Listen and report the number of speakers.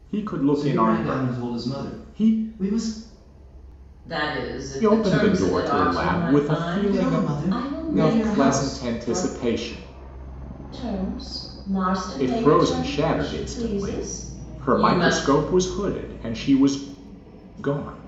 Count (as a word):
three